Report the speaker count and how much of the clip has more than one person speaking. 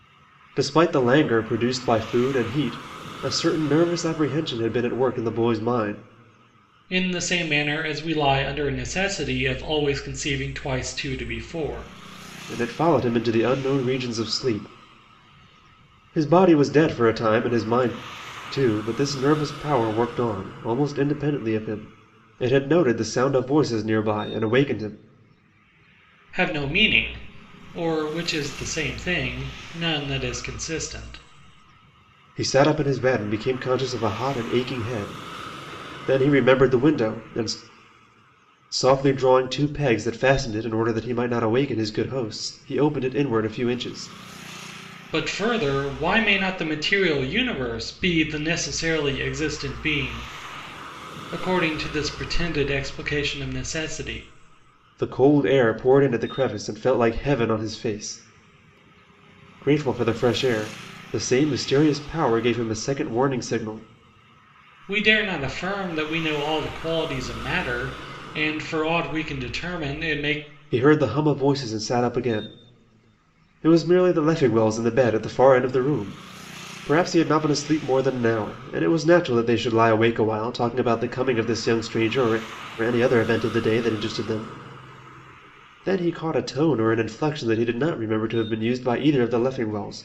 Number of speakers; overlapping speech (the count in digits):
2, no overlap